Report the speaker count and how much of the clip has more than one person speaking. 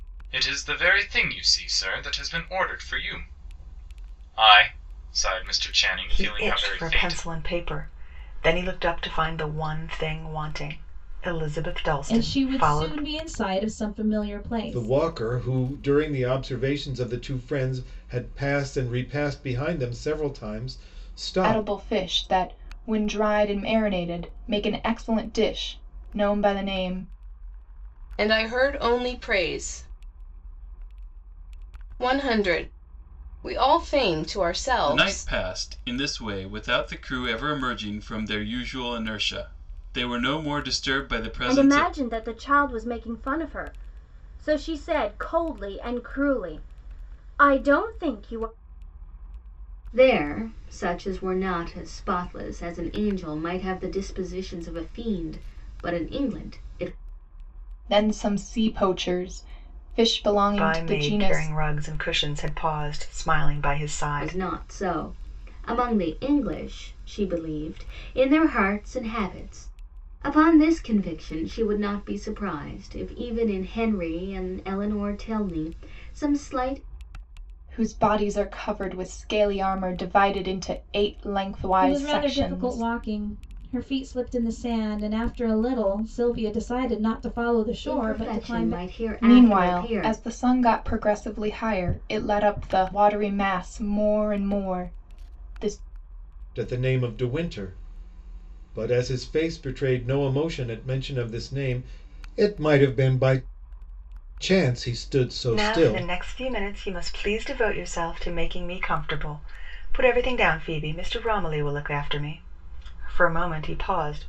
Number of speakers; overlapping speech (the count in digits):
9, about 8%